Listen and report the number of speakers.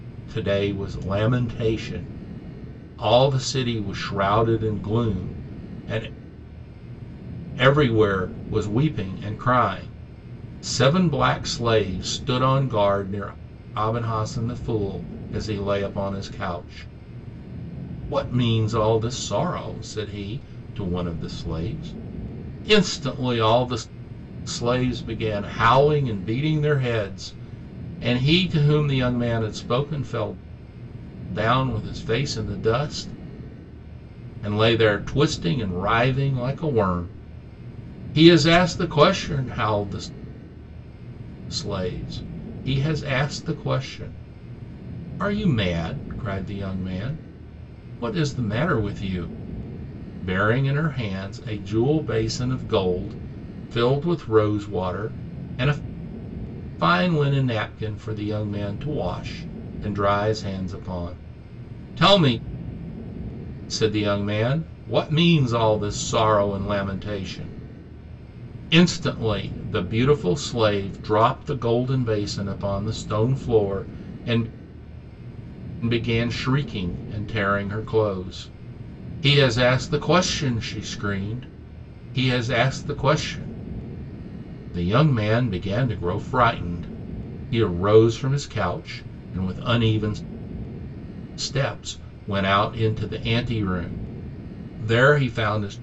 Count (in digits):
1